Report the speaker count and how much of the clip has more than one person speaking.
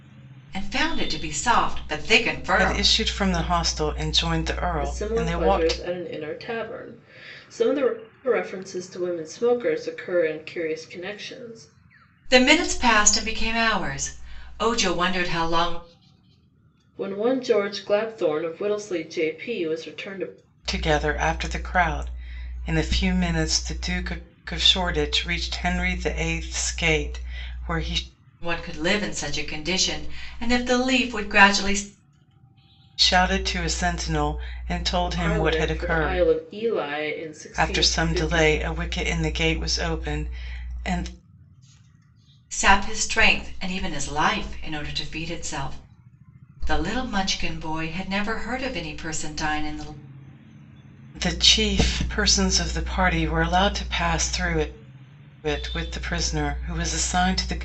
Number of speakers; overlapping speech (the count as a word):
three, about 6%